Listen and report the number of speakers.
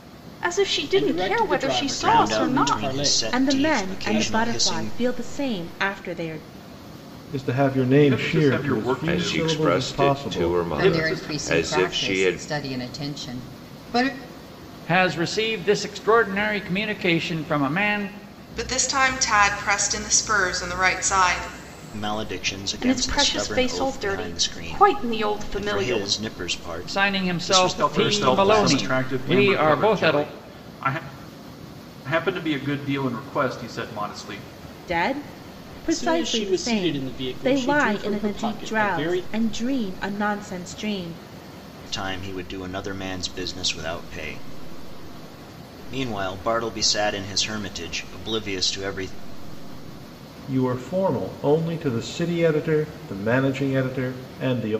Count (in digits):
10